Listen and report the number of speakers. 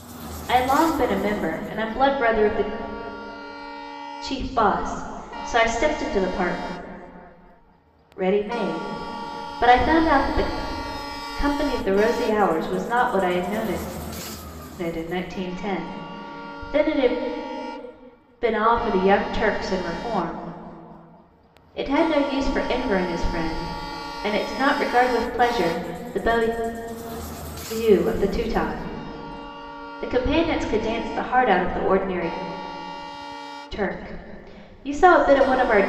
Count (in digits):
1